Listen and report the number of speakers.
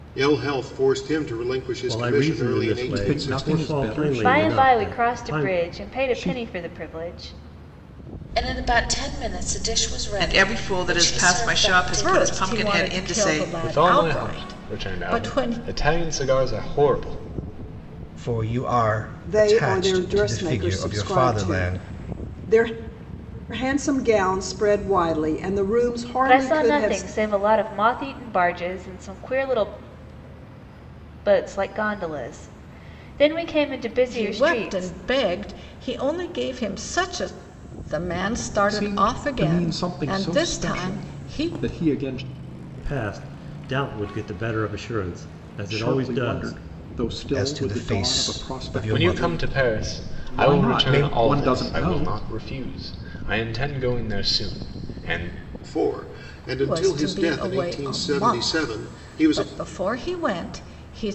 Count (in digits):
10